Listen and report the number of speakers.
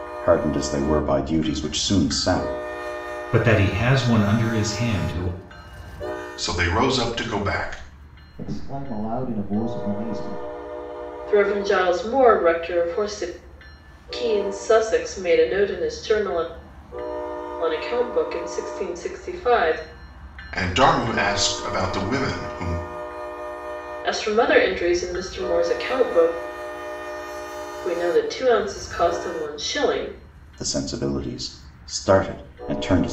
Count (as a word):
five